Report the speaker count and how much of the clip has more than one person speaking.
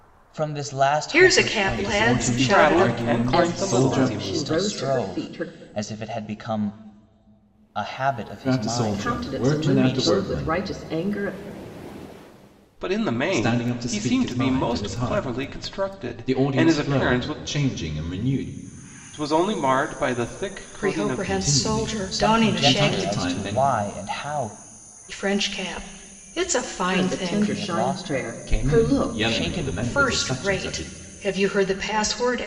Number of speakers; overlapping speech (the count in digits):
5, about 51%